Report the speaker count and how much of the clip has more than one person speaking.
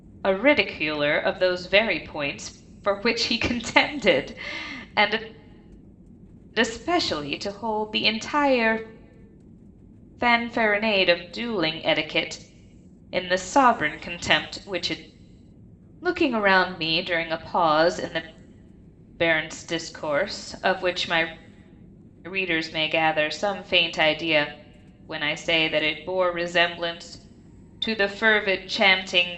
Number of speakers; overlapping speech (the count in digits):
1, no overlap